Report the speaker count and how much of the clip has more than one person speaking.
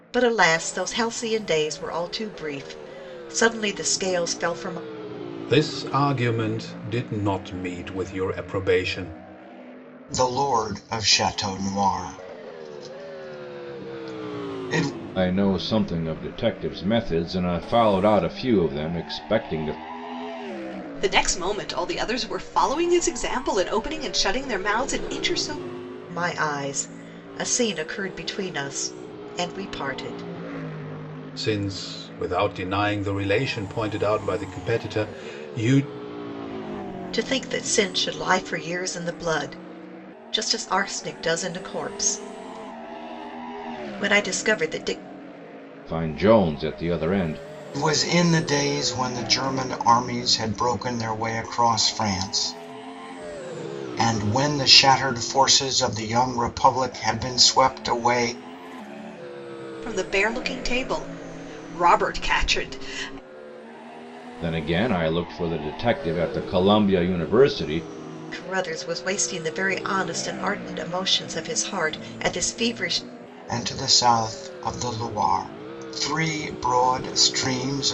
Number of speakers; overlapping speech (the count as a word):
five, no overlap